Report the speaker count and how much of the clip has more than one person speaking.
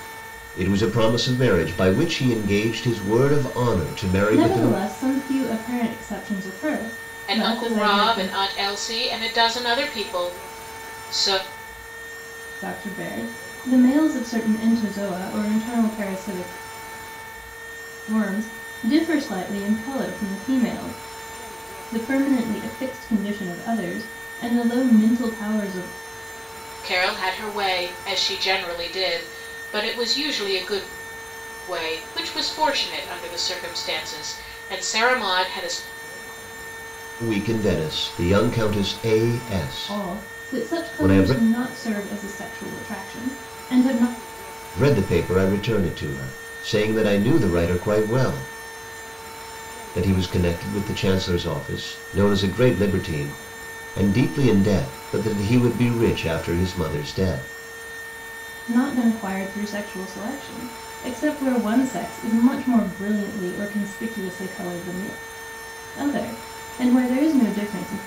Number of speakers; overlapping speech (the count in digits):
3, about 5%